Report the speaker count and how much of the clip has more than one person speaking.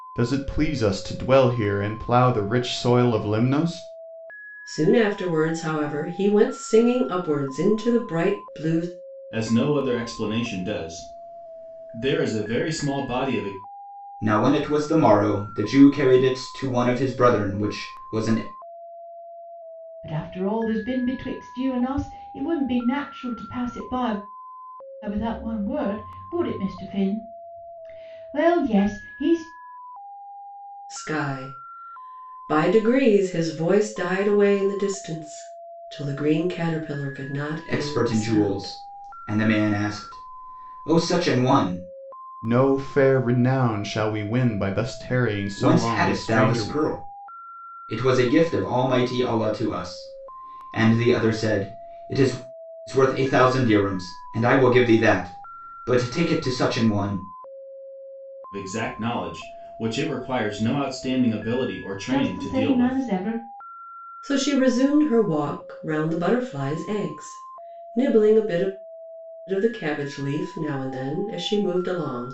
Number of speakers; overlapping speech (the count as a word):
five, about 5%